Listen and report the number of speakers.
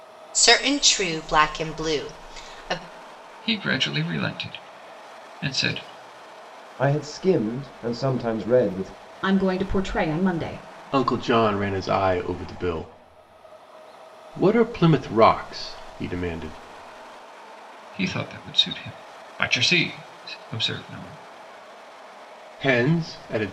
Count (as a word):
five